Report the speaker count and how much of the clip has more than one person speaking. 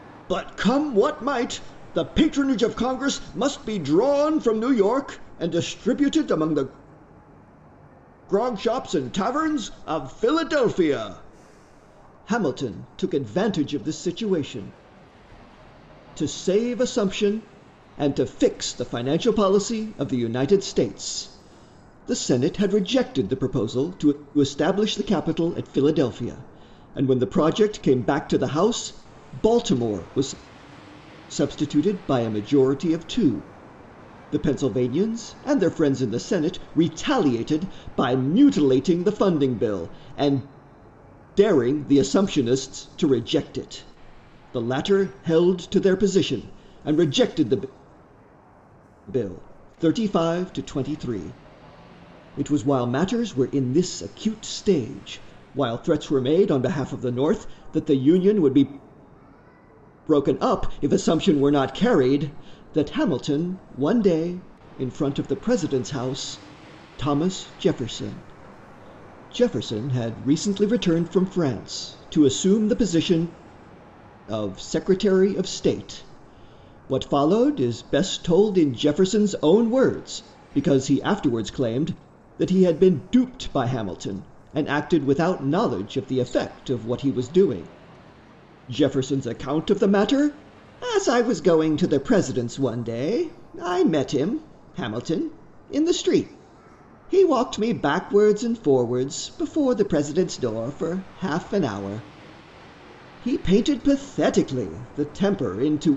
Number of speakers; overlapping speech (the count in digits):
1, no overlap